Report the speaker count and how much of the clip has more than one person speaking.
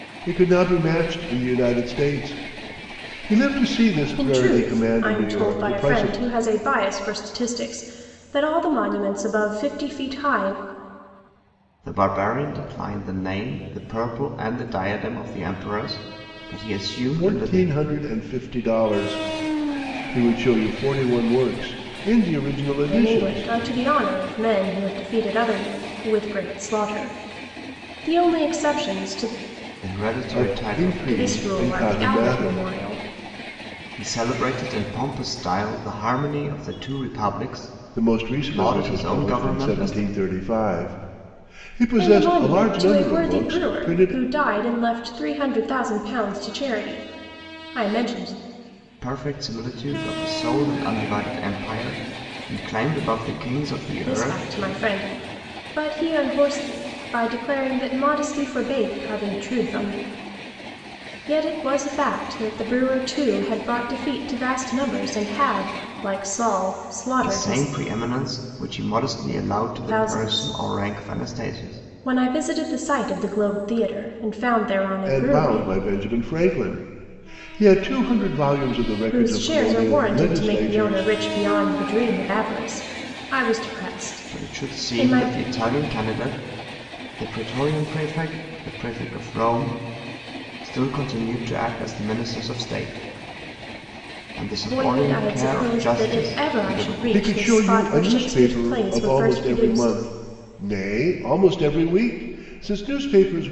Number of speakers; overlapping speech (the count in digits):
3, about 22%